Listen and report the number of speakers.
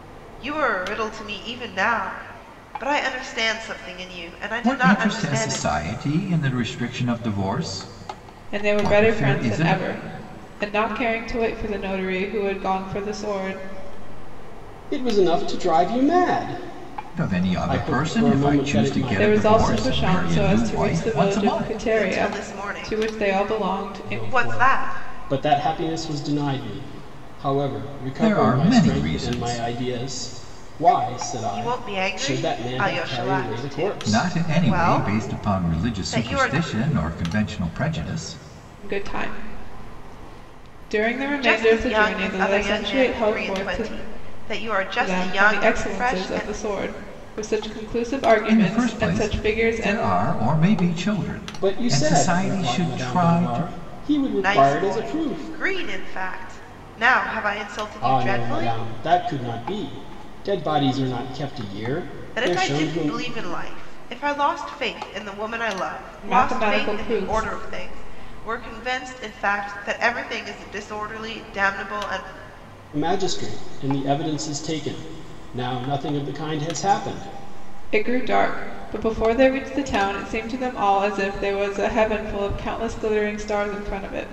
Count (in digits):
4